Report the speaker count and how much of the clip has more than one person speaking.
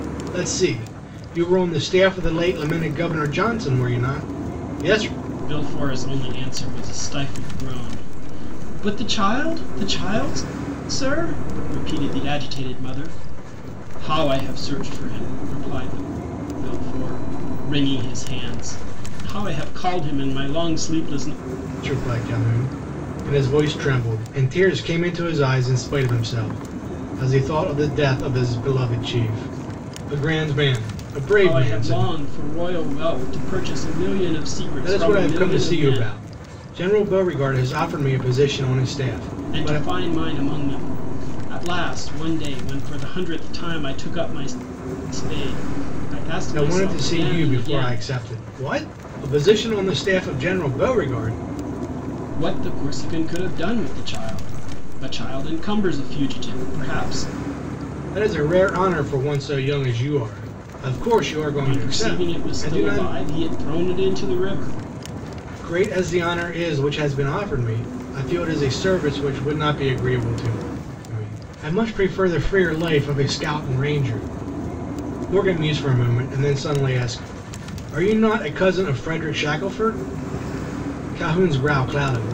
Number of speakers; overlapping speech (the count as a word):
two, about 7%